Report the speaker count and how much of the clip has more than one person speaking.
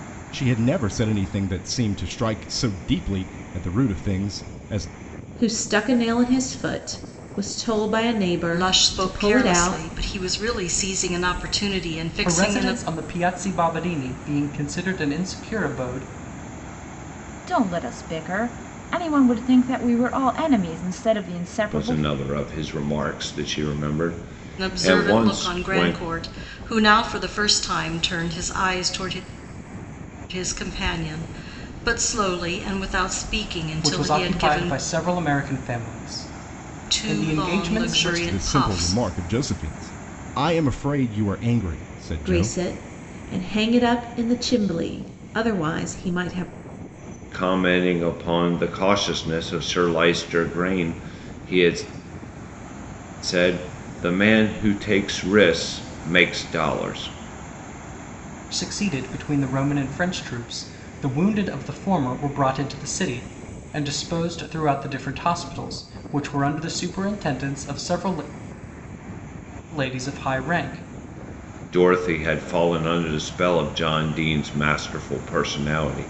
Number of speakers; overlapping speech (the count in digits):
6, about 10%